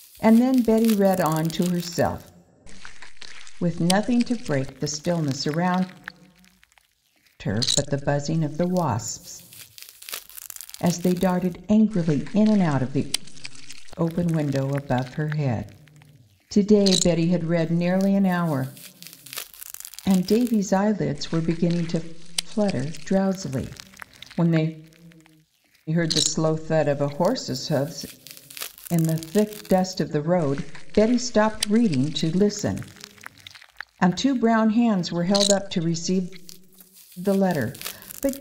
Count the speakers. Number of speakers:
1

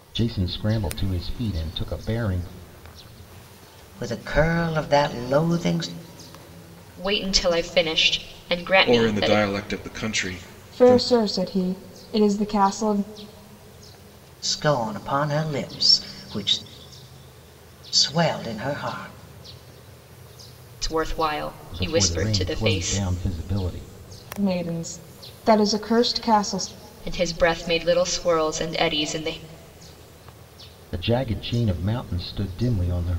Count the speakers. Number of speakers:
5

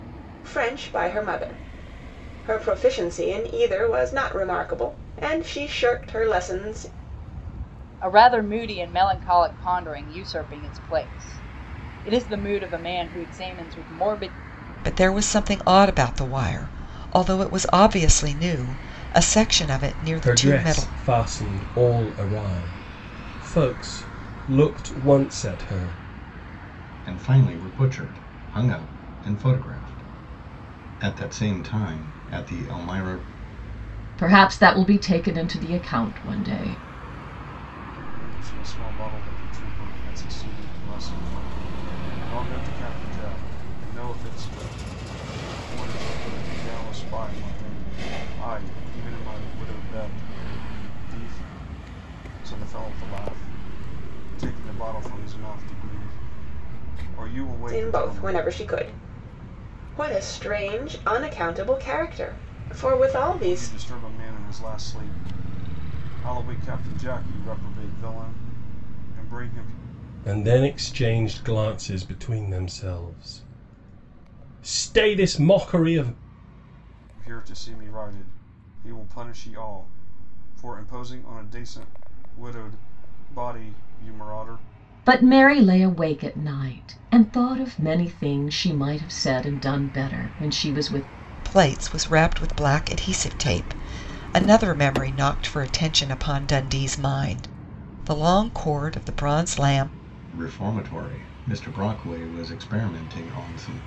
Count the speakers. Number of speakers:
7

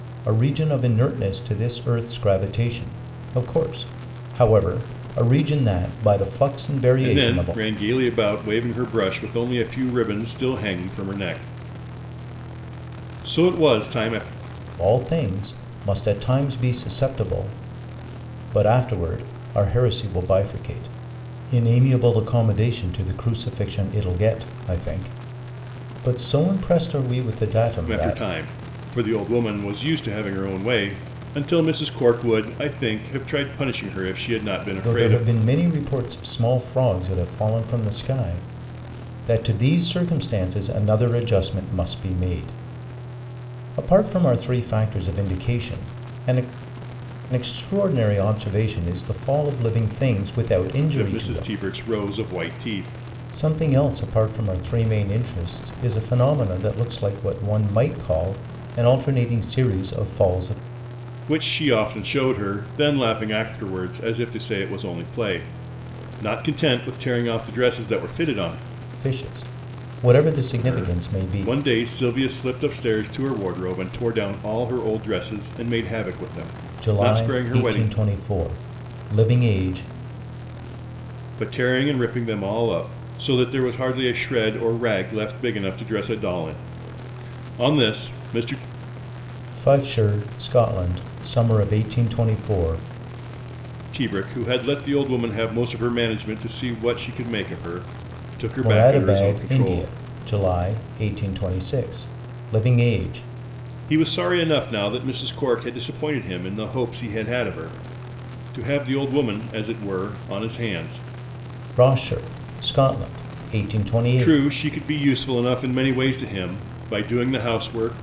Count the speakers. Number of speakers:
2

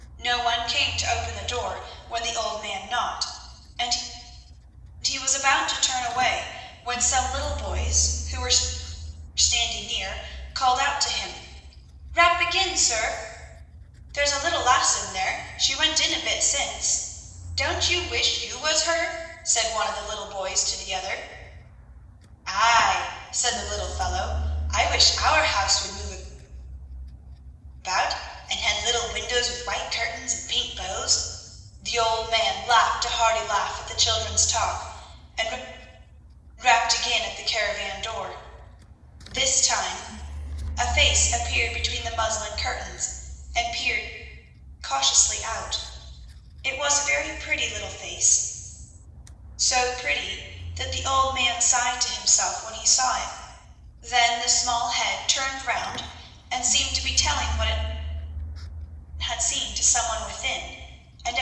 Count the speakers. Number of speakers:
1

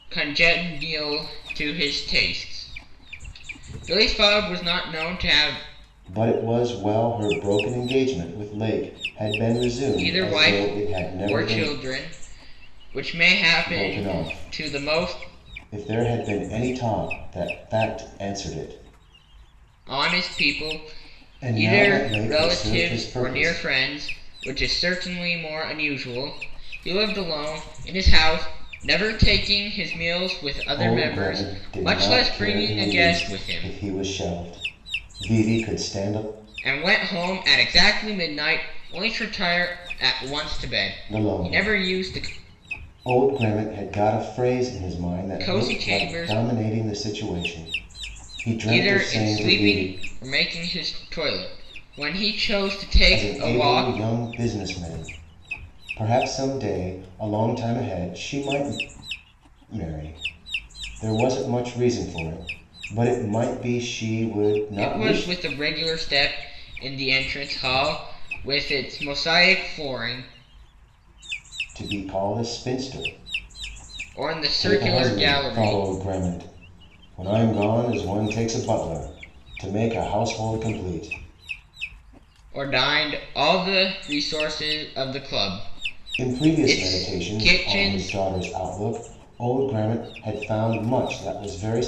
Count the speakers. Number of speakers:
2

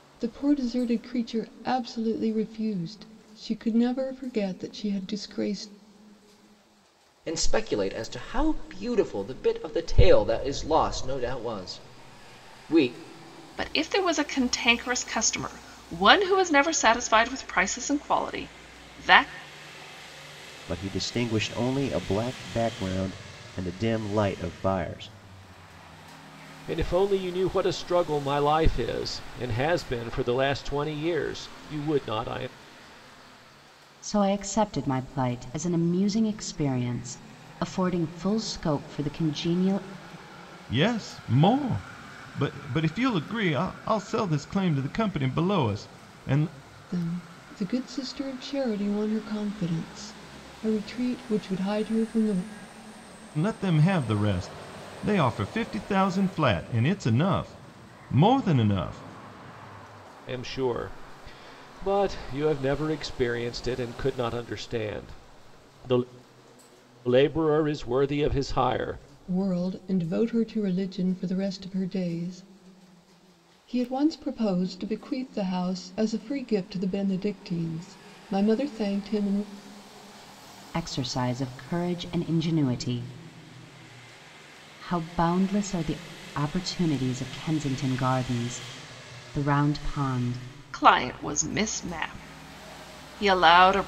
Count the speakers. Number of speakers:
7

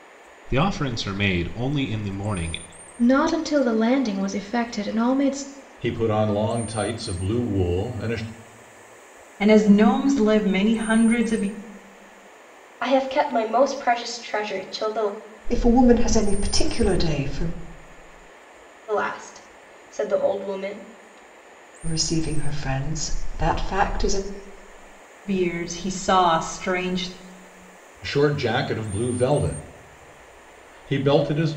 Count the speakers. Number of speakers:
6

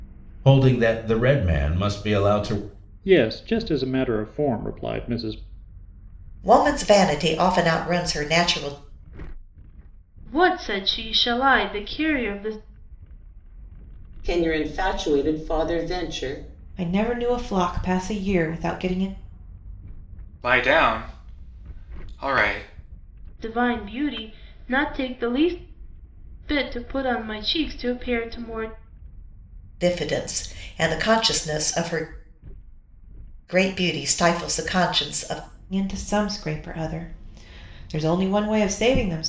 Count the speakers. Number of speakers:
7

